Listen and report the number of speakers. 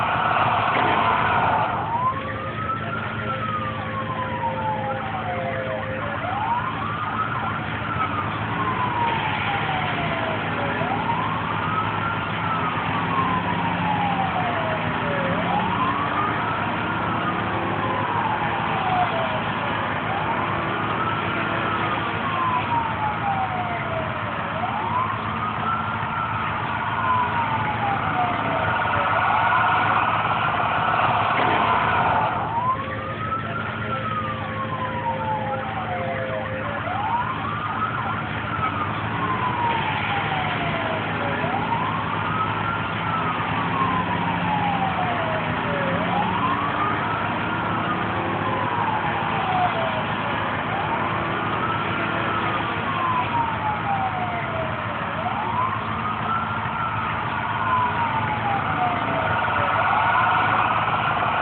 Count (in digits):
0